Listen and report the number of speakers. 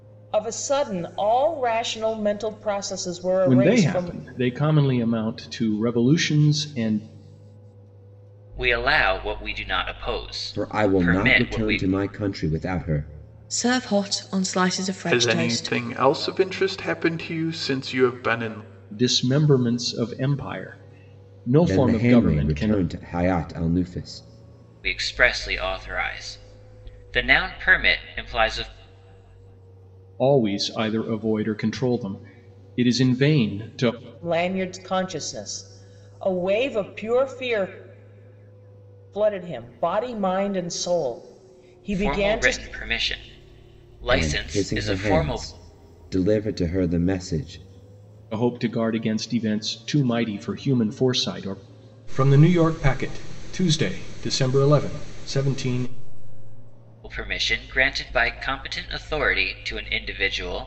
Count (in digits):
6